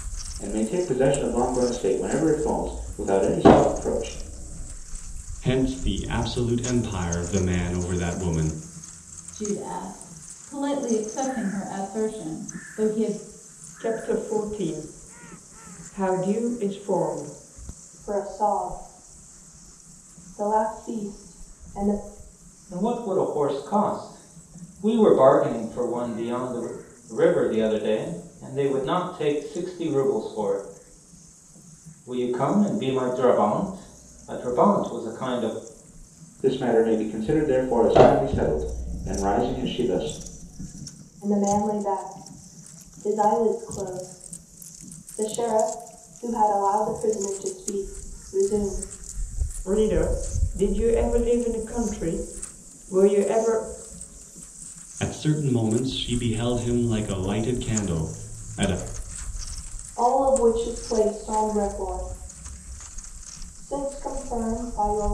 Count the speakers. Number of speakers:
six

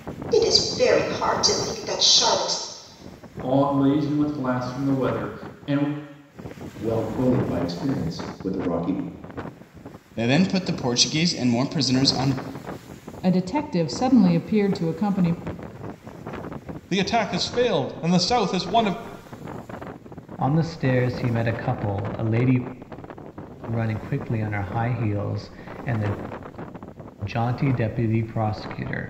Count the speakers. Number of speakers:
seven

